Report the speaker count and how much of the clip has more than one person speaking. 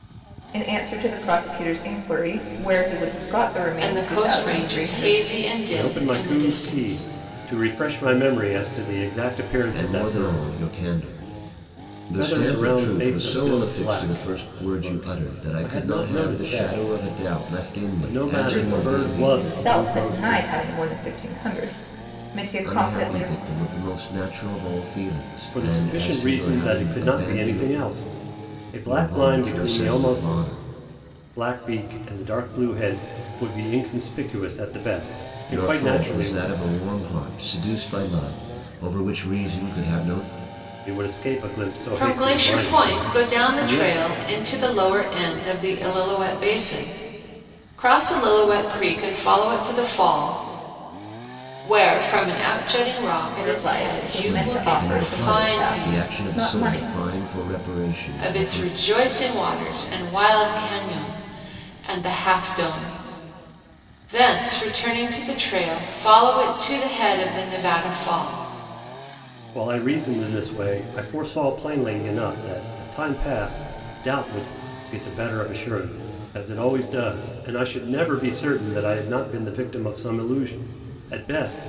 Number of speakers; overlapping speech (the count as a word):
four, about 28%